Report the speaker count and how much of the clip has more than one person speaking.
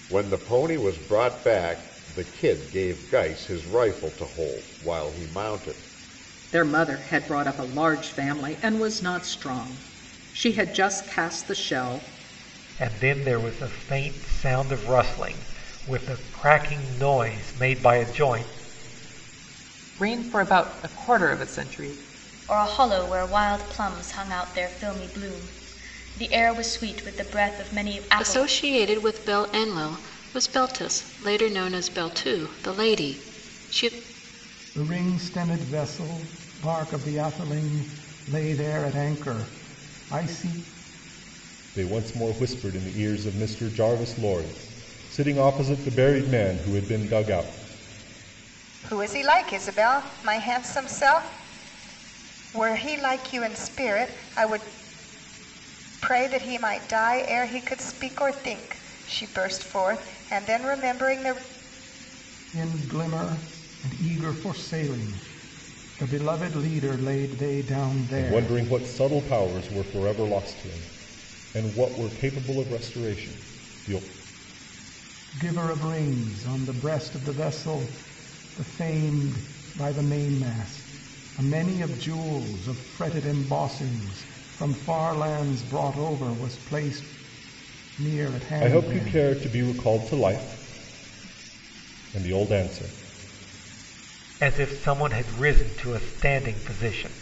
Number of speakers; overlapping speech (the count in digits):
9, about 1%